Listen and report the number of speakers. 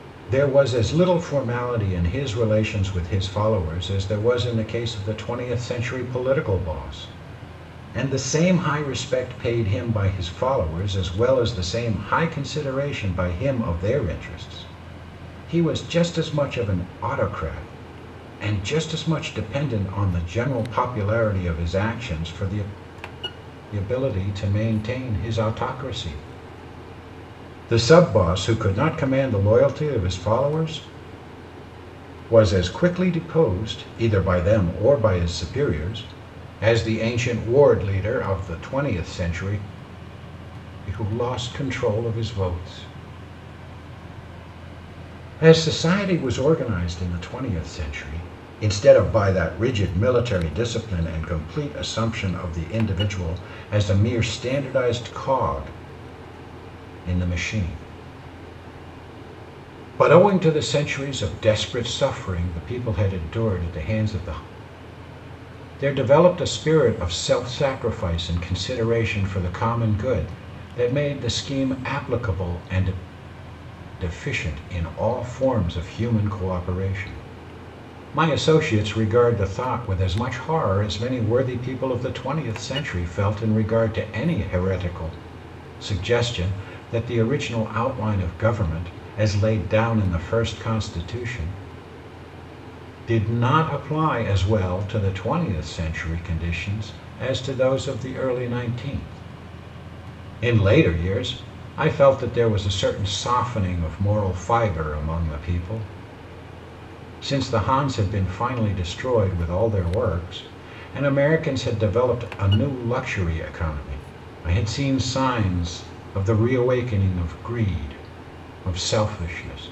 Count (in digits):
1